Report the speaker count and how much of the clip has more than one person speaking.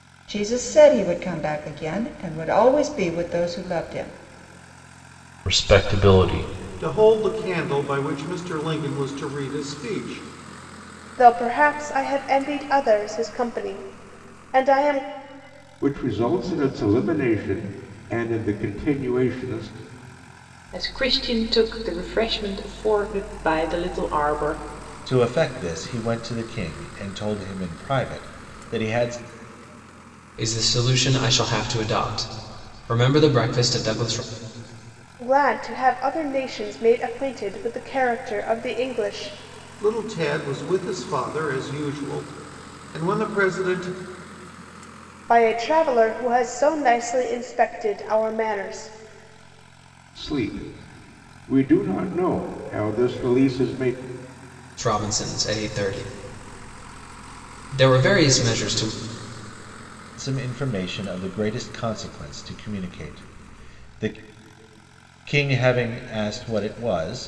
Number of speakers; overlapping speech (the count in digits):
8, no overlap